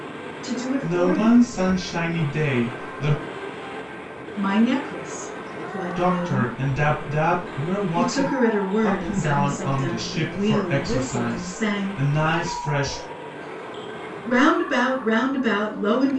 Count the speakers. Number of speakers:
2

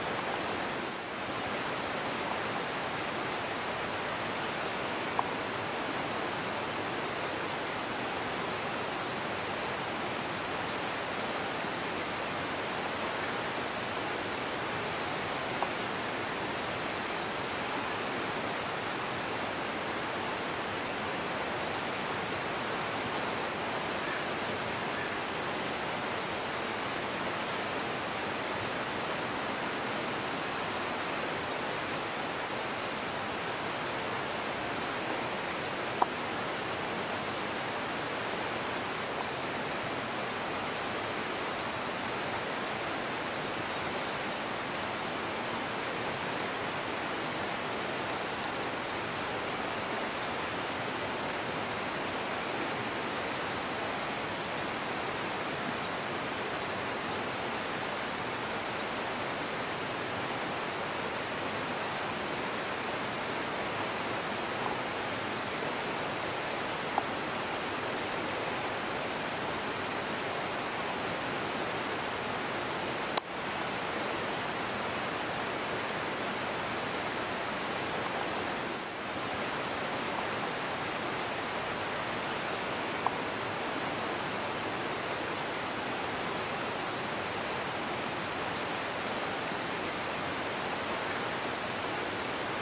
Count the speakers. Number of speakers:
0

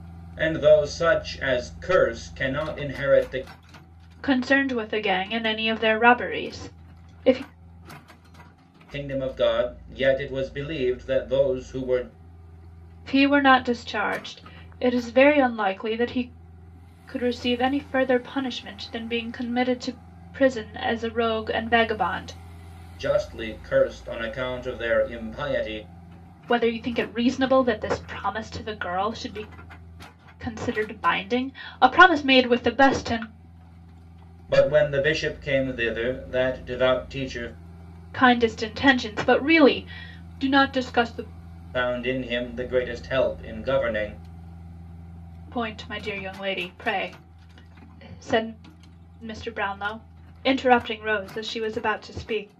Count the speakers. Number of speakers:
2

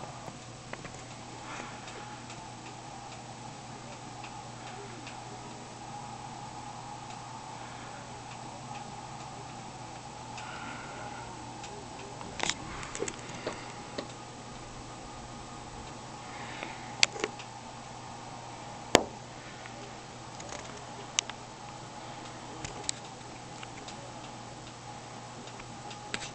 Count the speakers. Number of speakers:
0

